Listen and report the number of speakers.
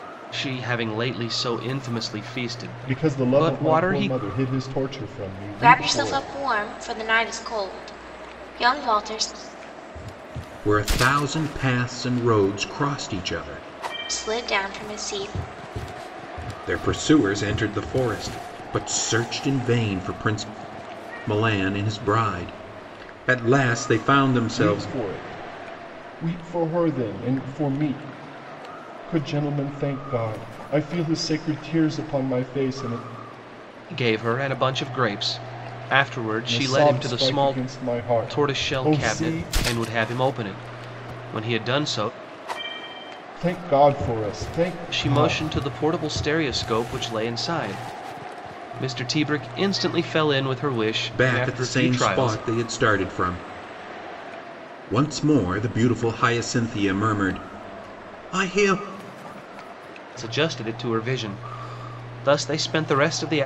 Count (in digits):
4